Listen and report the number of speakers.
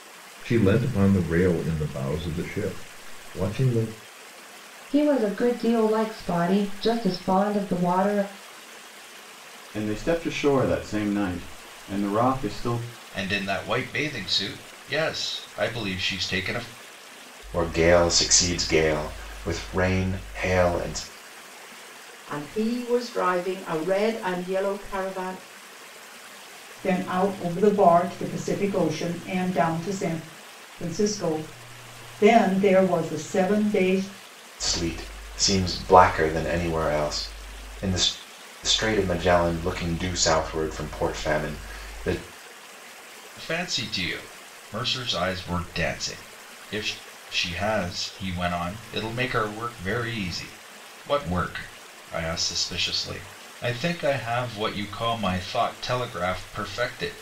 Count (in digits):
7